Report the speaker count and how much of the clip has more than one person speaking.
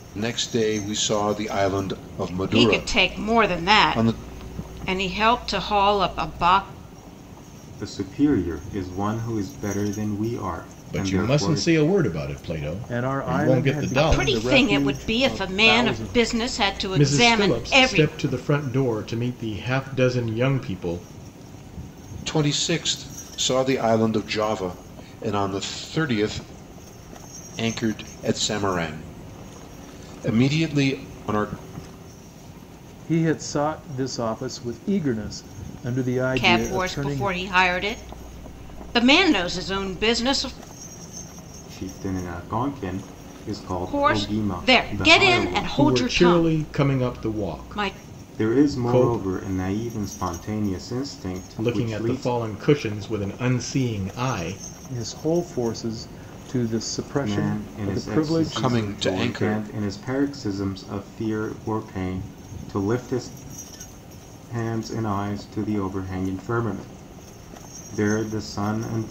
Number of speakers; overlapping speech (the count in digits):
5, about 24%